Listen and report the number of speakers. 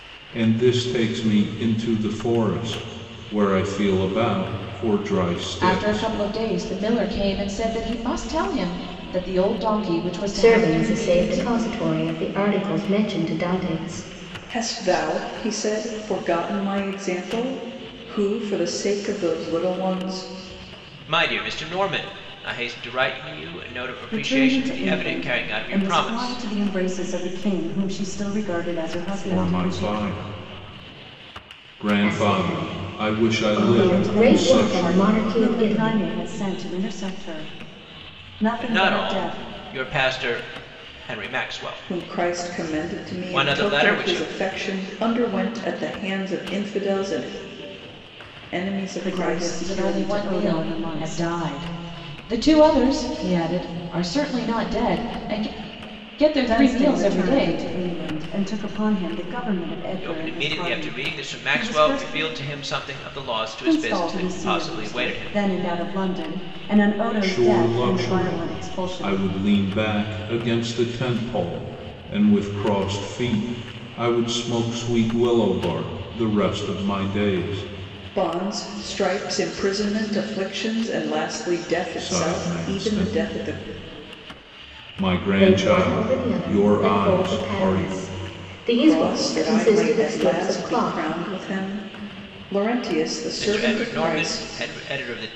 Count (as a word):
six